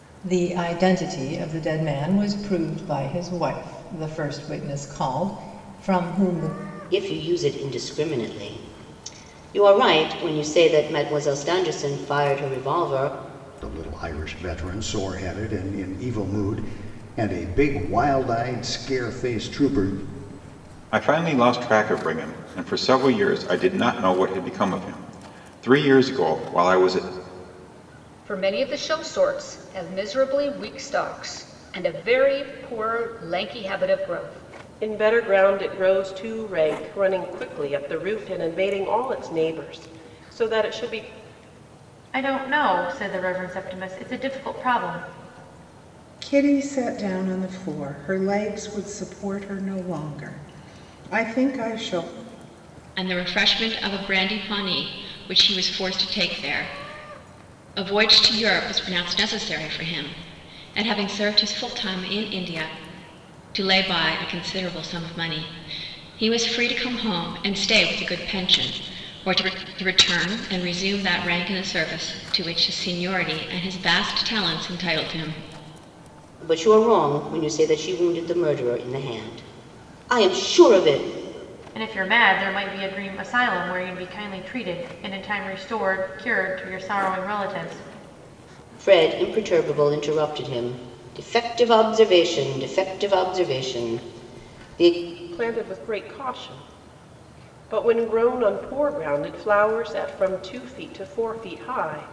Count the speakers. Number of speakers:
nine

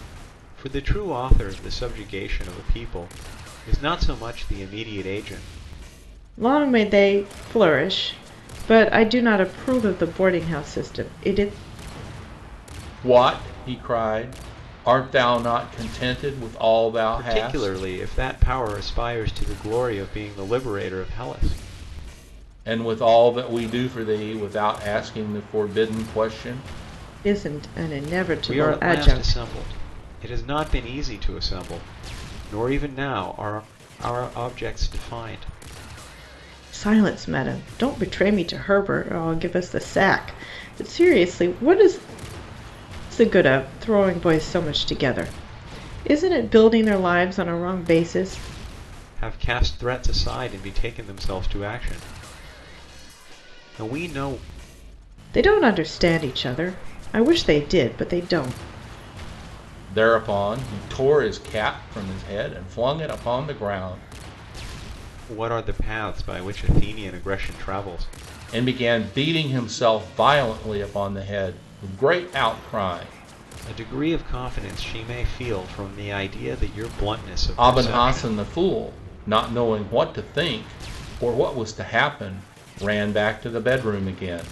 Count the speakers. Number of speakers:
three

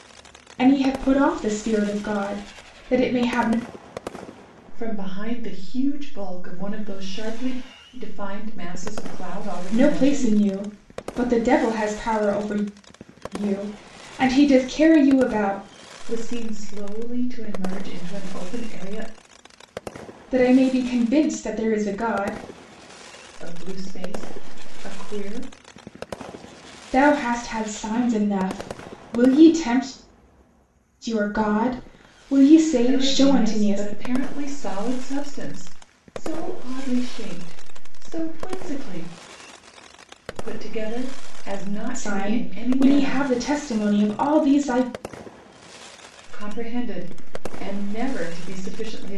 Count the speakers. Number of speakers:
two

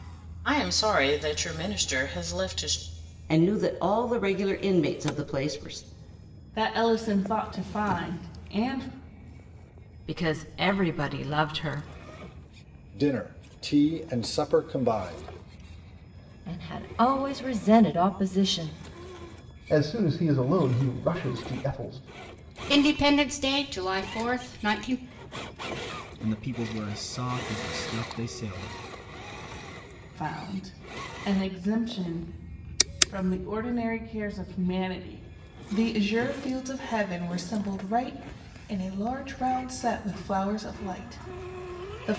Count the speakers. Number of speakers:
nine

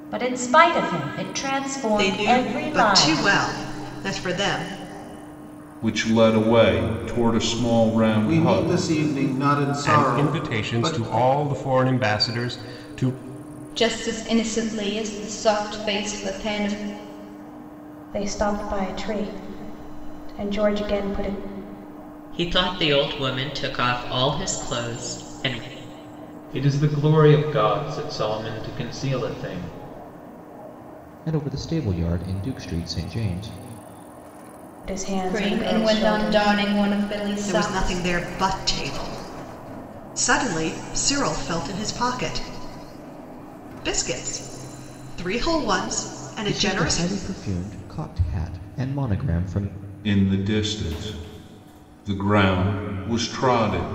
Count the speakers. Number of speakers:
ten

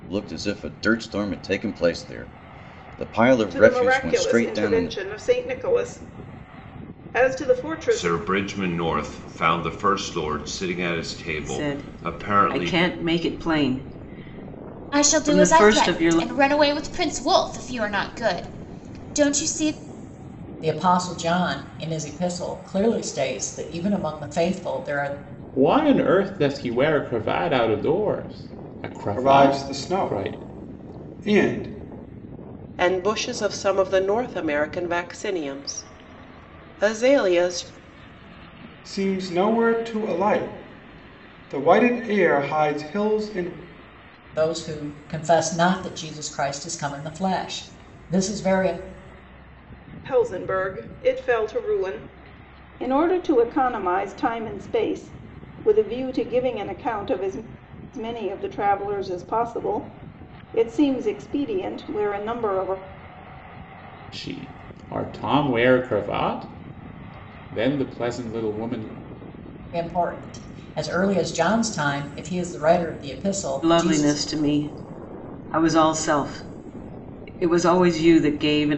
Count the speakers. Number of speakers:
nine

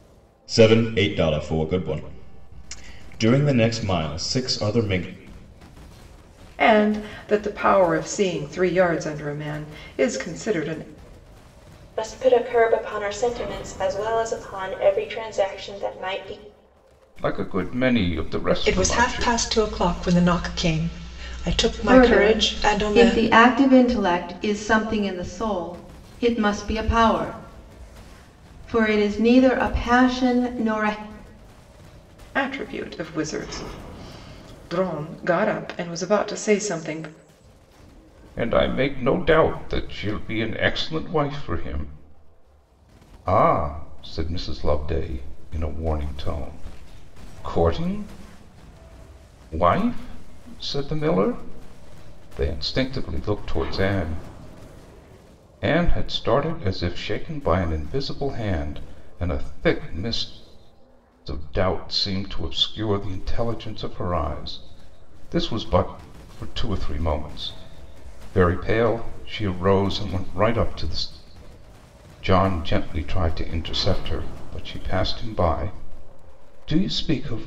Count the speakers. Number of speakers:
six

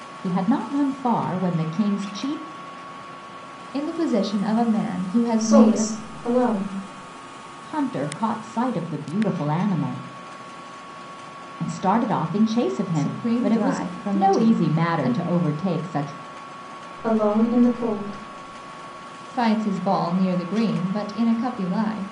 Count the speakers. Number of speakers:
three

